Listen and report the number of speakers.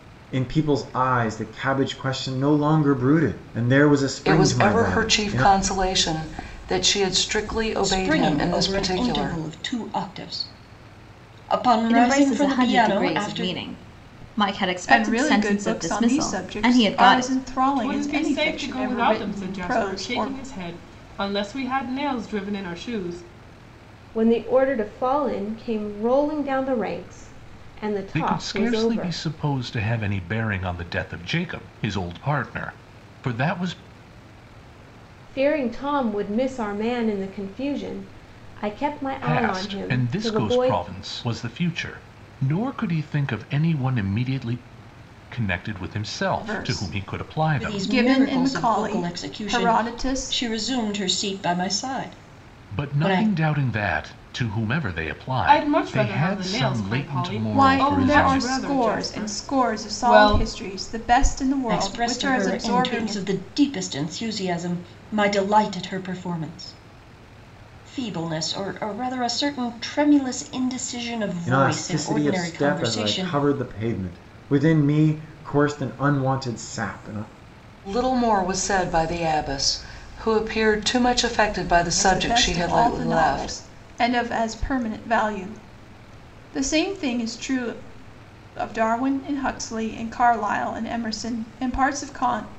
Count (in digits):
8